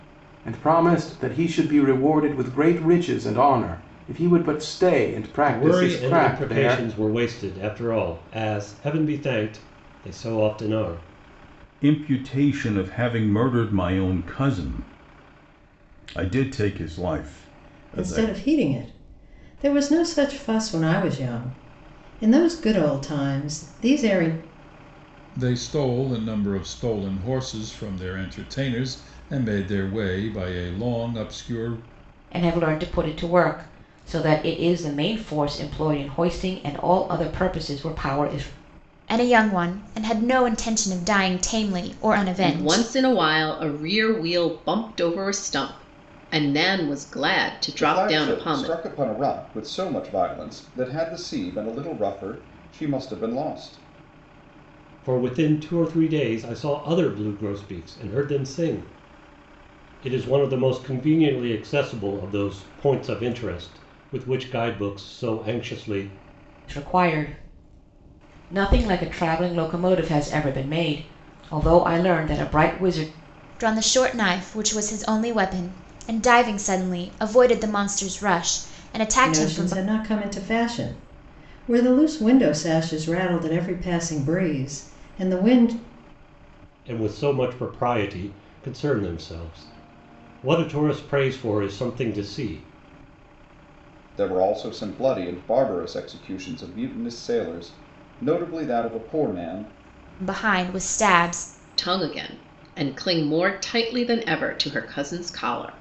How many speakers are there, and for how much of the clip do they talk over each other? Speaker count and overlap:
nine, about 4%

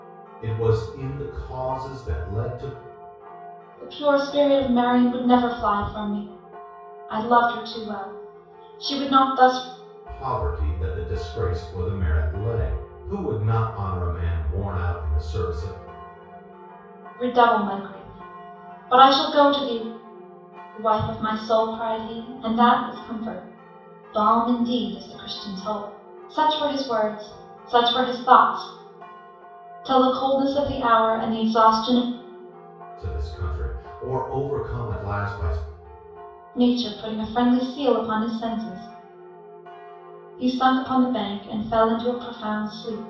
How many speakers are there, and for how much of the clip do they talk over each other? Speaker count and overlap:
two, no overlap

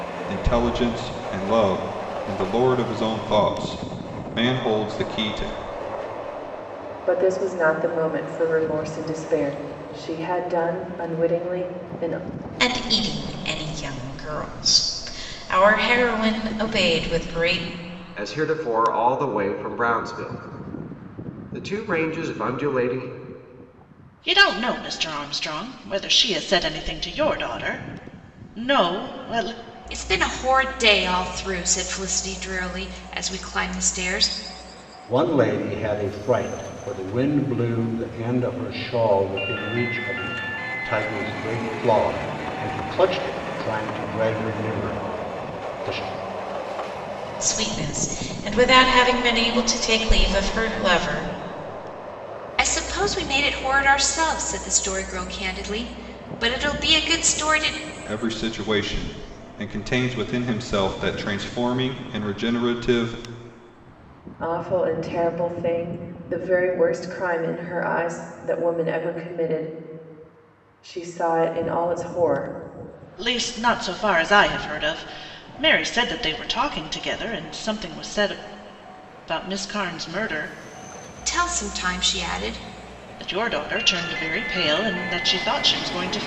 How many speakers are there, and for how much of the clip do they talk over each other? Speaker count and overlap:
seven, no overlap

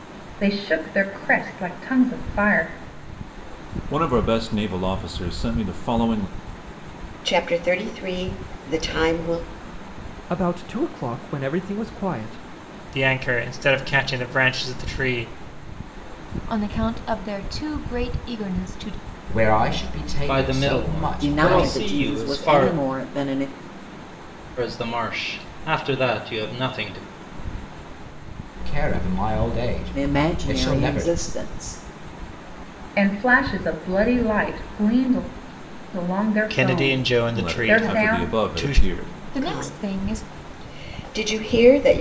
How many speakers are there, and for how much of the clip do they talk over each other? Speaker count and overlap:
nine, about 18%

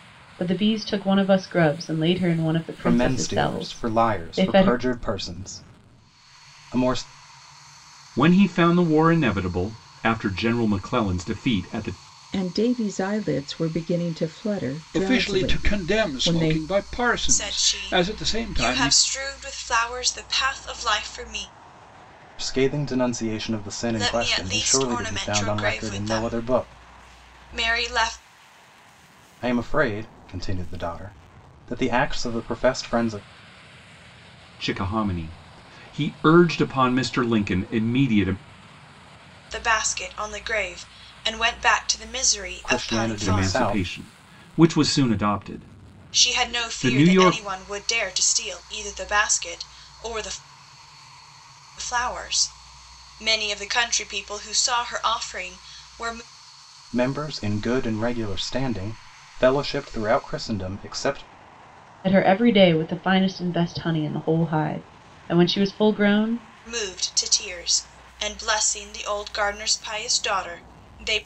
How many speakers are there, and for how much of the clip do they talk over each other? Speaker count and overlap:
six, about 15%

